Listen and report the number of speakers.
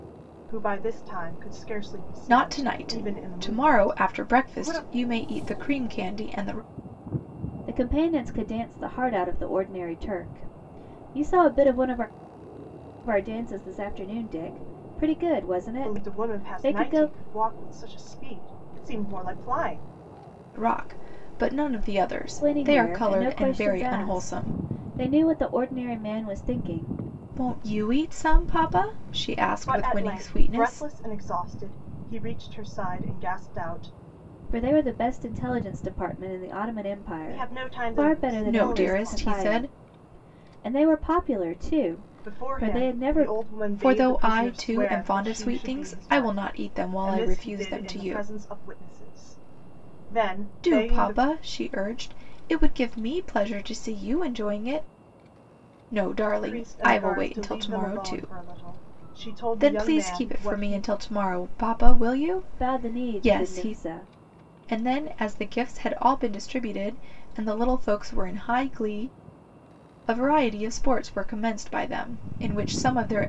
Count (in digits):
3